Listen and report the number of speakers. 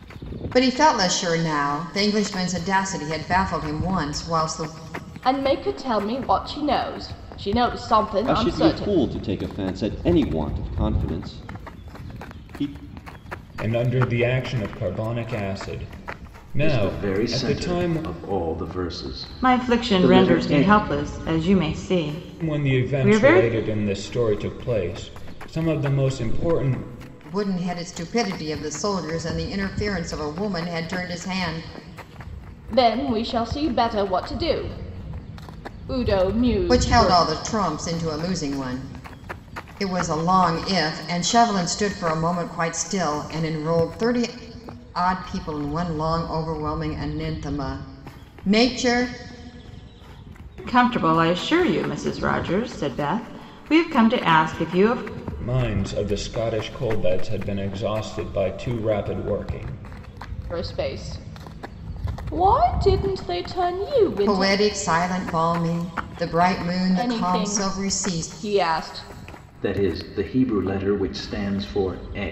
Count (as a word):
six